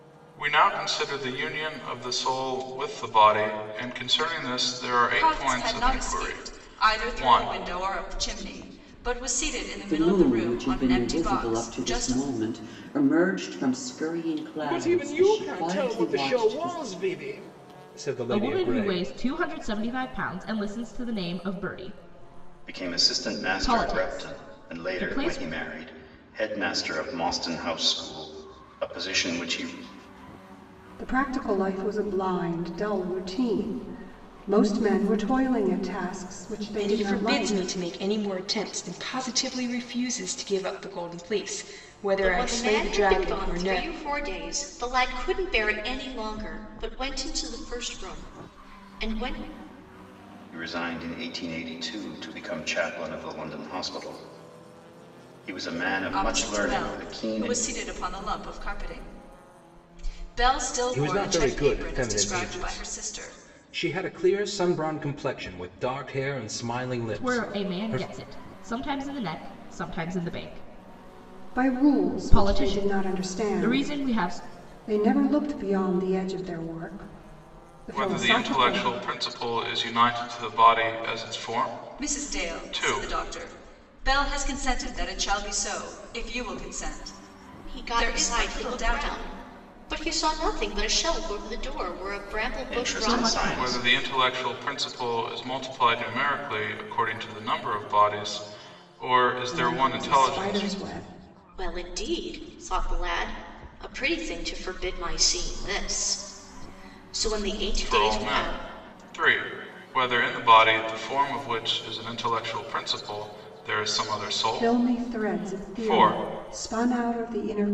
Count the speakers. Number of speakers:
nine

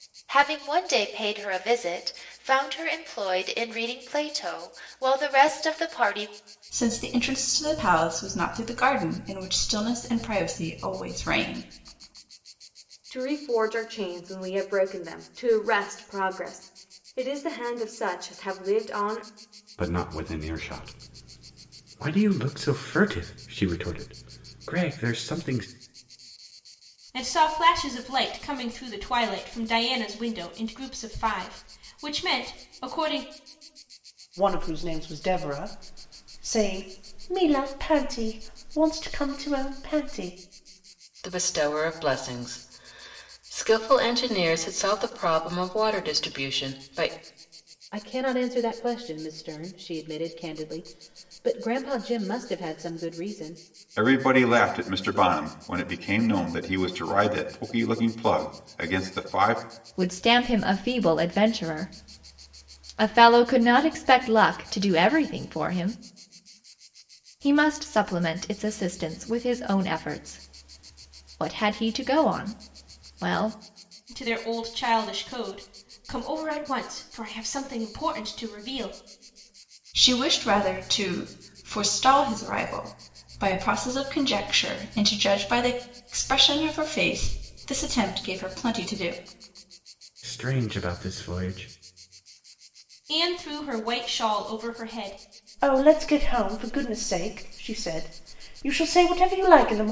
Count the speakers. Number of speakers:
ten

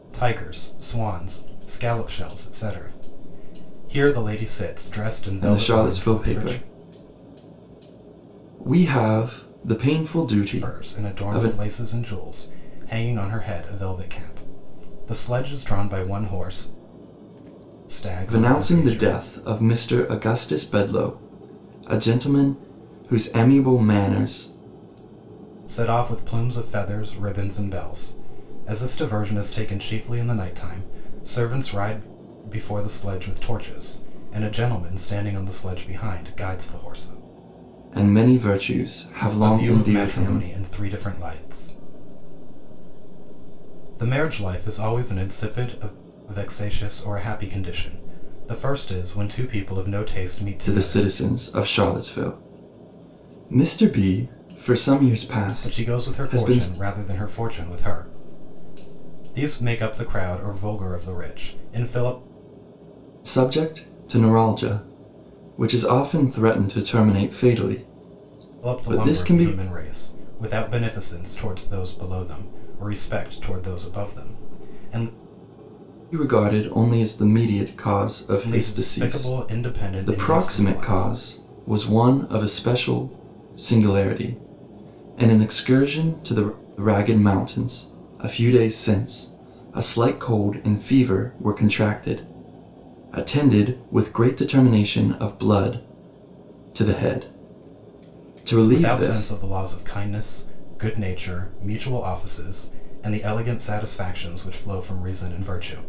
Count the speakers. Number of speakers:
two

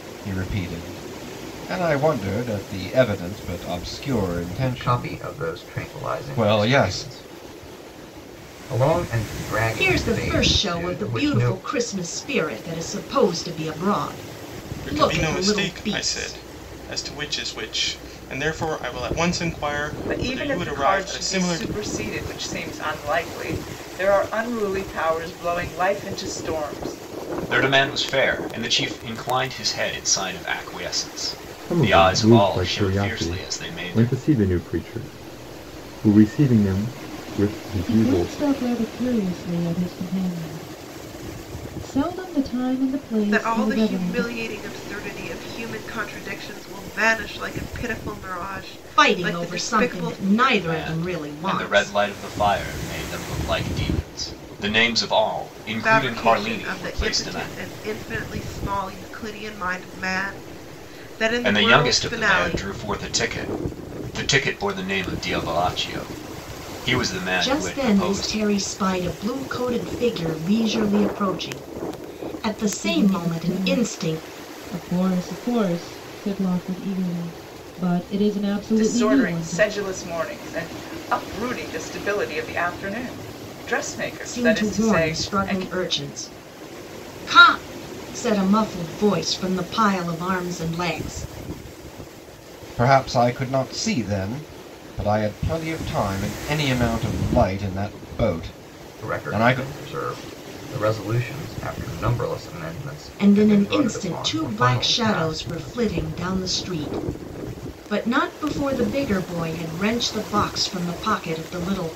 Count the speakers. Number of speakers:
nine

